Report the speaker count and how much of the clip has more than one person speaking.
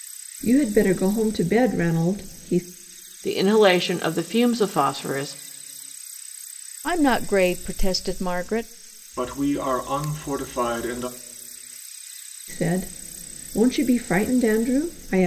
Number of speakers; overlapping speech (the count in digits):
4, no overlap